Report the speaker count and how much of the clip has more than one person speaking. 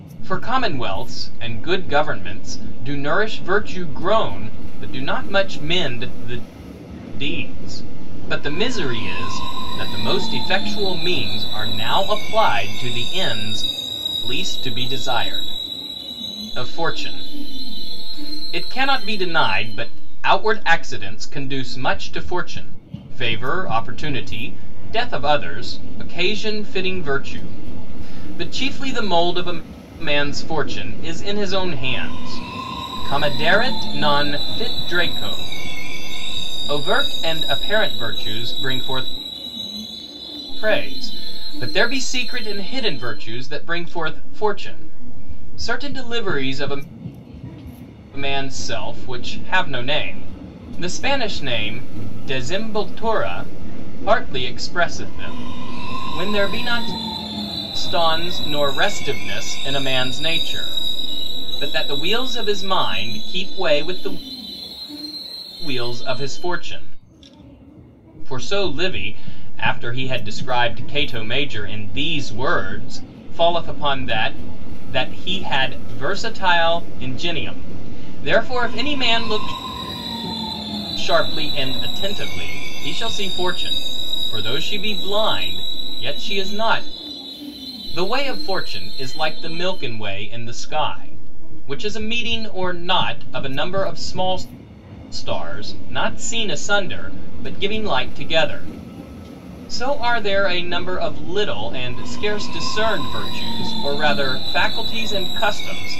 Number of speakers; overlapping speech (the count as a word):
one, no overlap